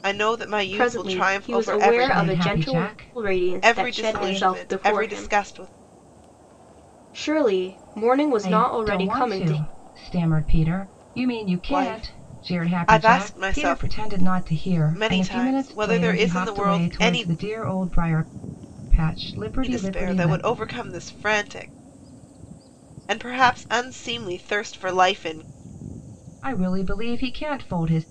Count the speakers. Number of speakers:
3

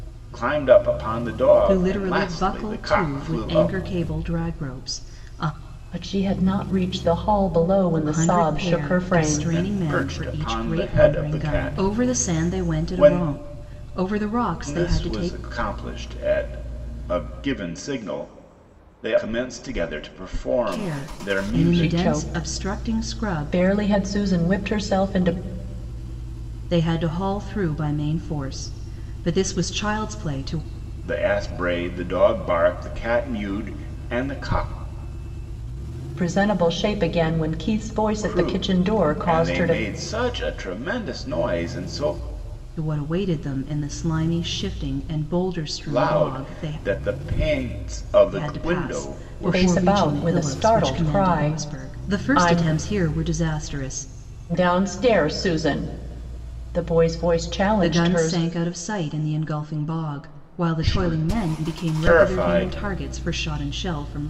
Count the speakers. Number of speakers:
3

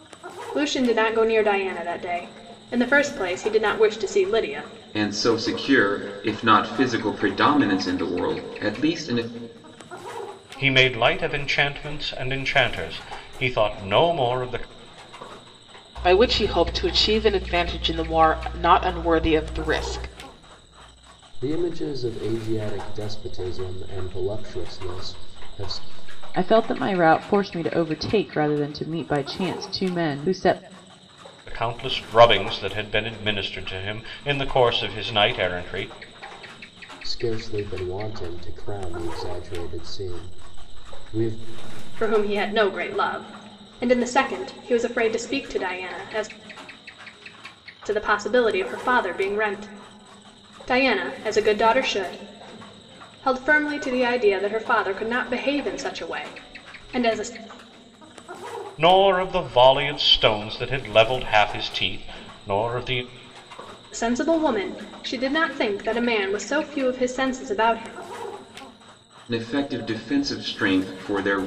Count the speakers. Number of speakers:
6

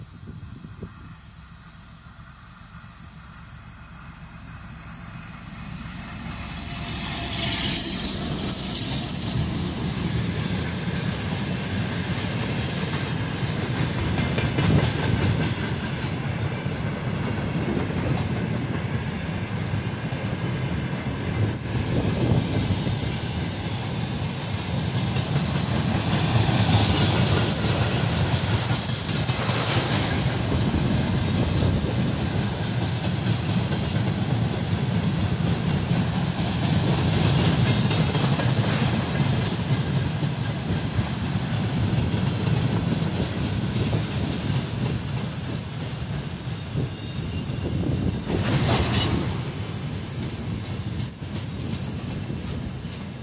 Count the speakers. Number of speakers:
0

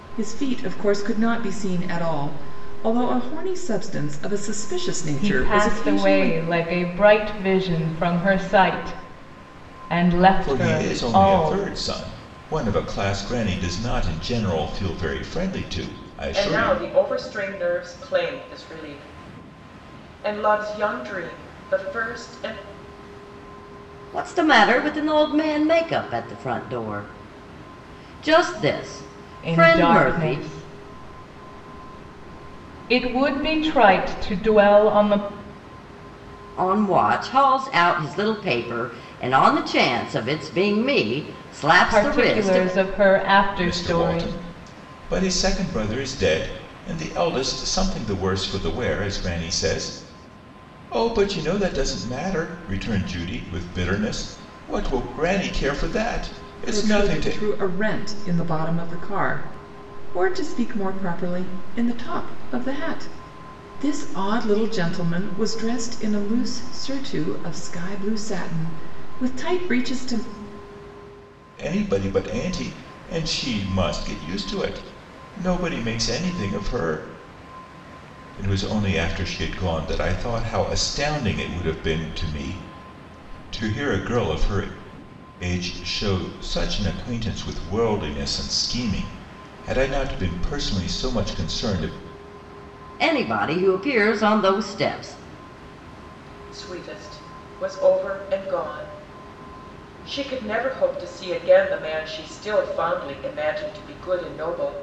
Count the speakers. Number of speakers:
5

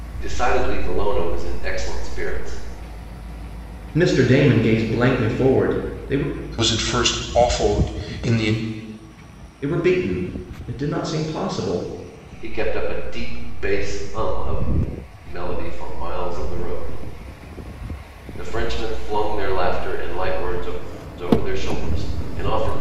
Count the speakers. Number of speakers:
3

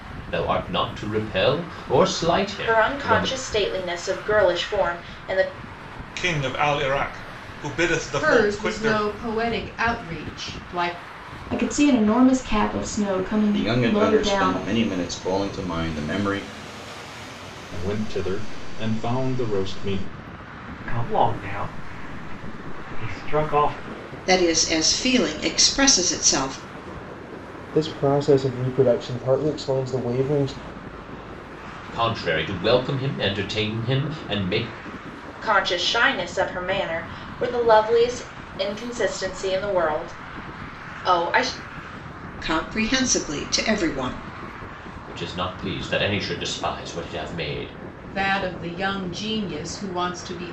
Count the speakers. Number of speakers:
10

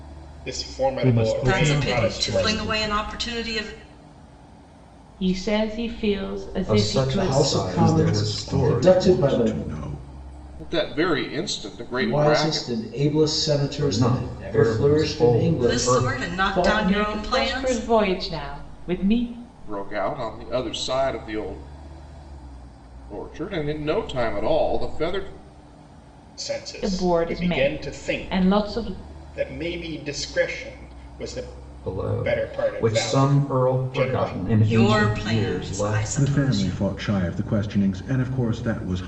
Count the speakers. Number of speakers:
8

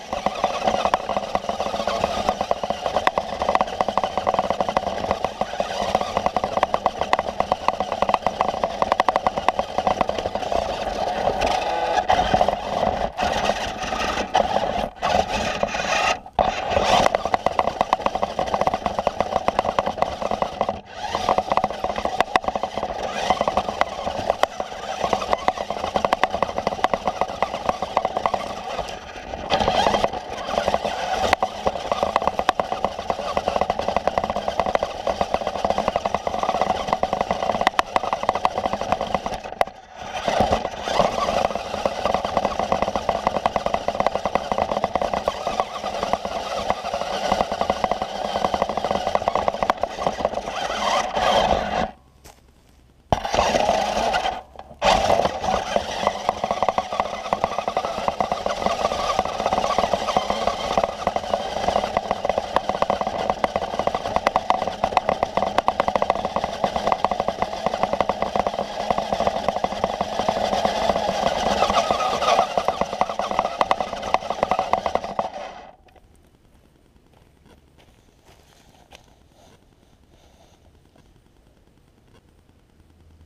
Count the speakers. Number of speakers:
0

